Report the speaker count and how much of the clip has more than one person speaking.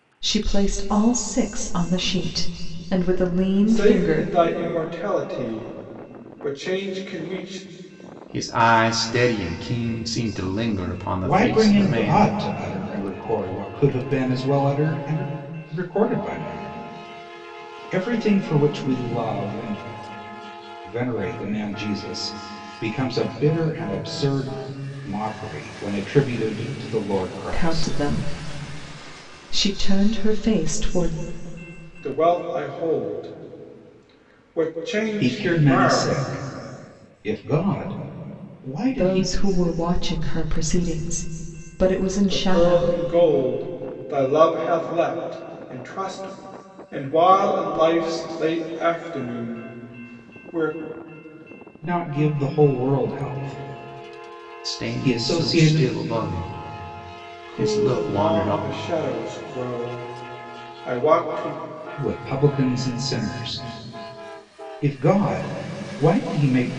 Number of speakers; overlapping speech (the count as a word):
four, about 10%